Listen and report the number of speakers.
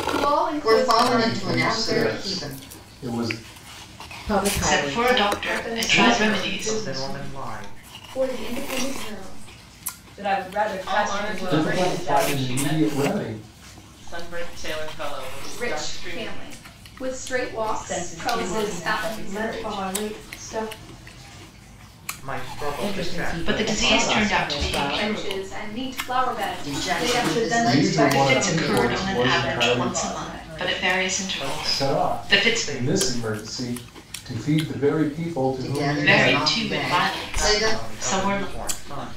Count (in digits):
10